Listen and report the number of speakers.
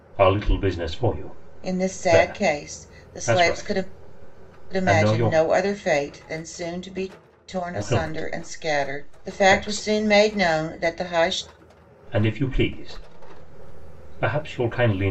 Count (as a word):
two